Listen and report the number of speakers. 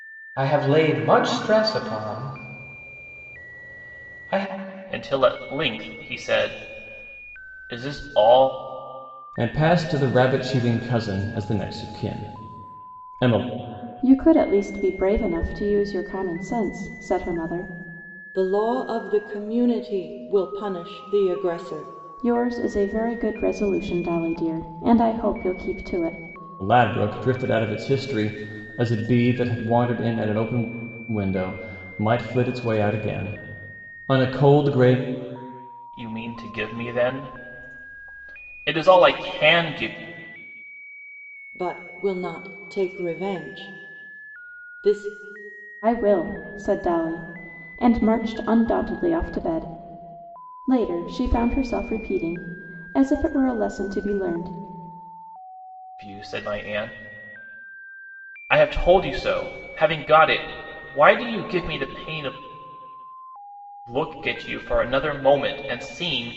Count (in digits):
5